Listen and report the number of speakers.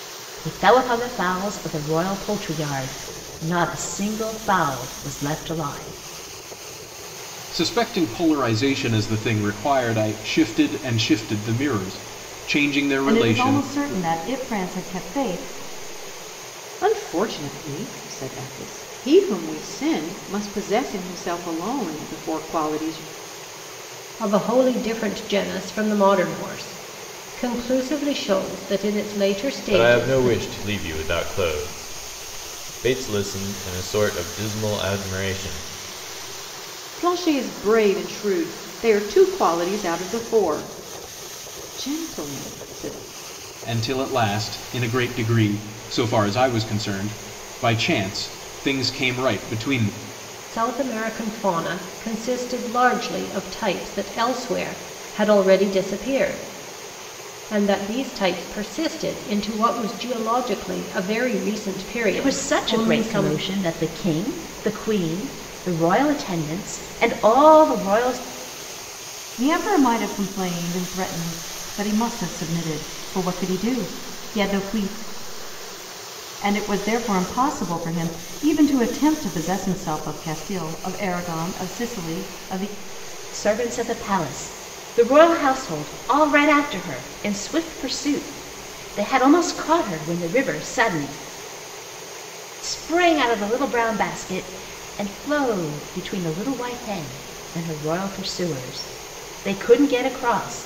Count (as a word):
six